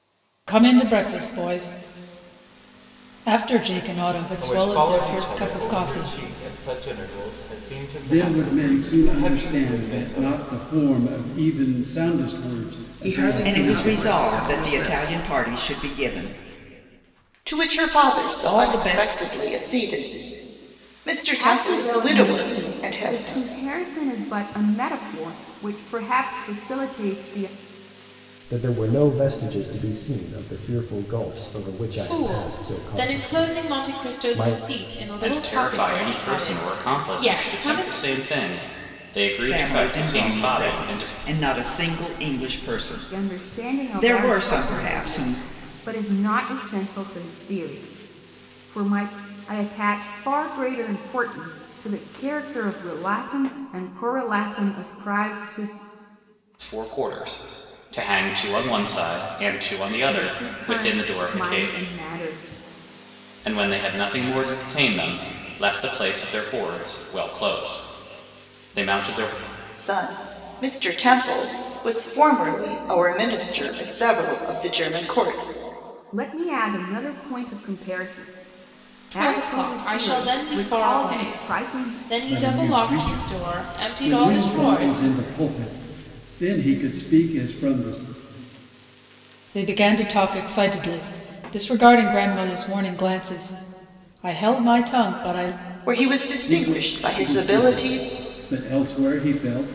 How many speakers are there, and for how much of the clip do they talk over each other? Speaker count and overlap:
ten, about 29%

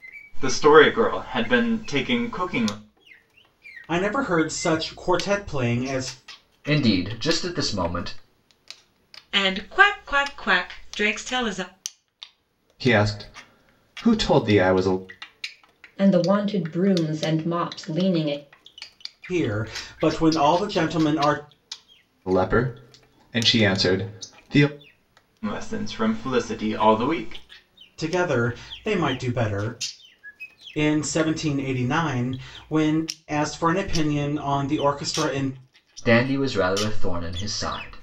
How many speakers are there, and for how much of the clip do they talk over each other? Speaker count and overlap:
six, no overlap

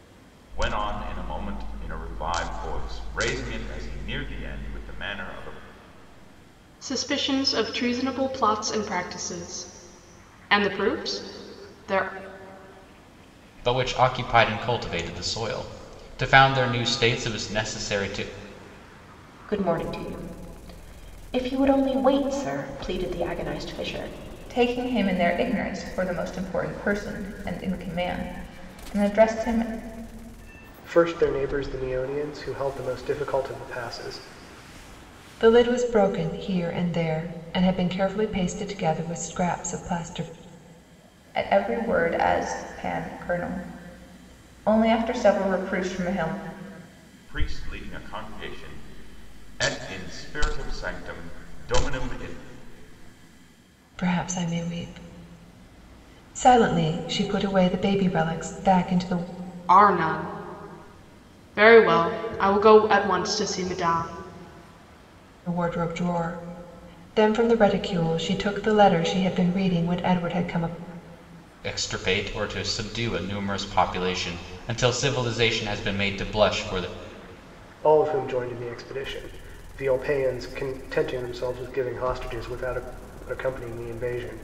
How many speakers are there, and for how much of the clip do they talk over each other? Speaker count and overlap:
seven, no overlap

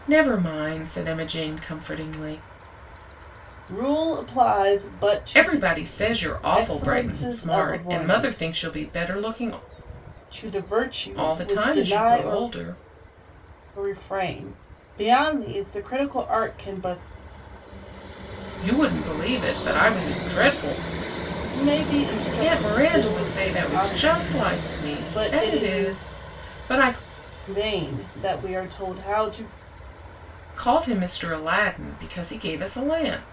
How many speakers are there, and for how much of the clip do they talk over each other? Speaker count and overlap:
two, about 21%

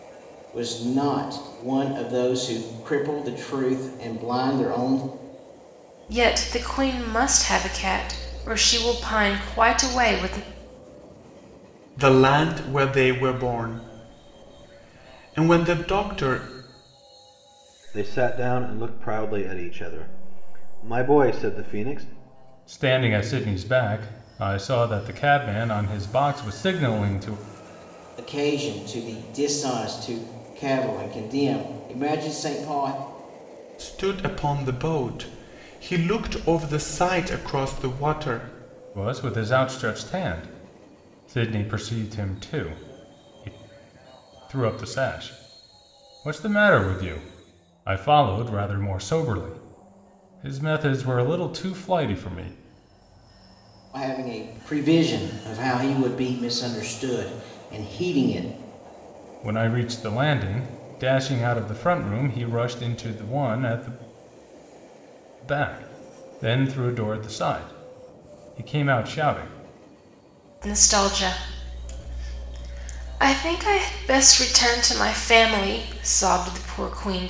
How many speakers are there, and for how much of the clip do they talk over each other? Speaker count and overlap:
five, no overlap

